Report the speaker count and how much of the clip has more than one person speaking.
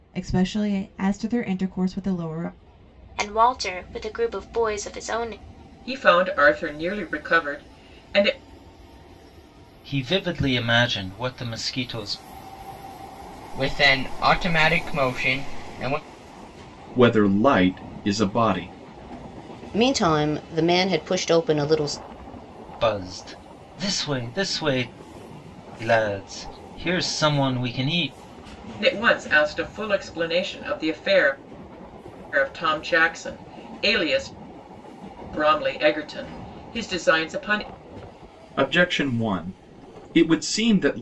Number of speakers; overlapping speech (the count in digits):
7, no overlap